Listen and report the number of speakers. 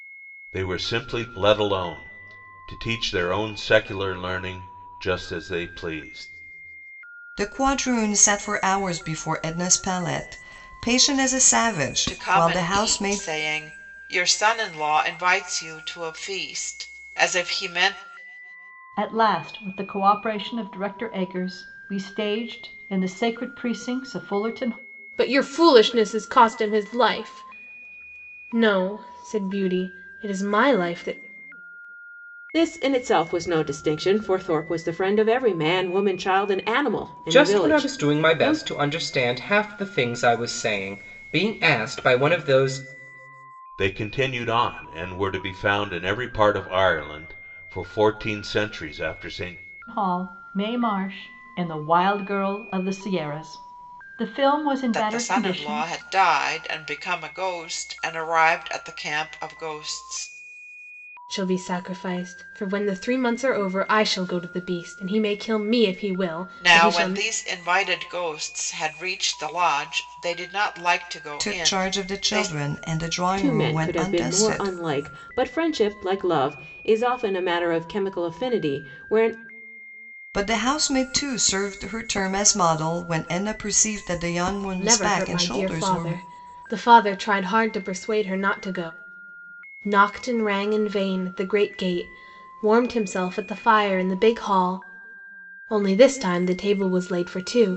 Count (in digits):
7